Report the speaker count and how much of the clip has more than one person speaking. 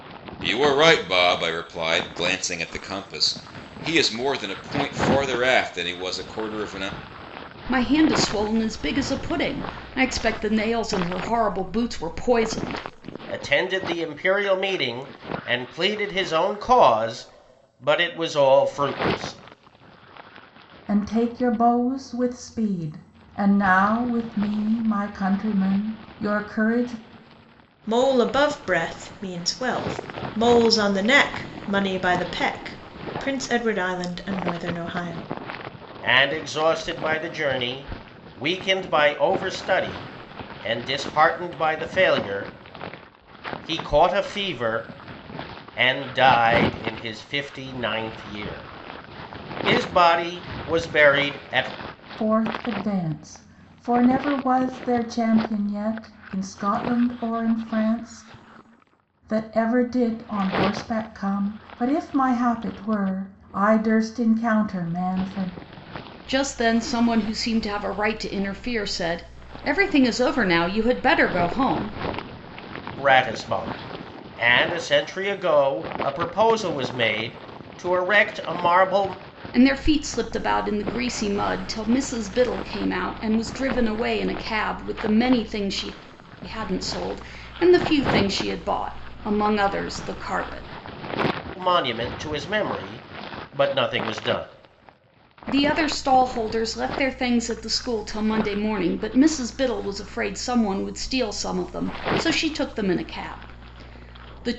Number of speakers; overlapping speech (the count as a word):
five, no overlap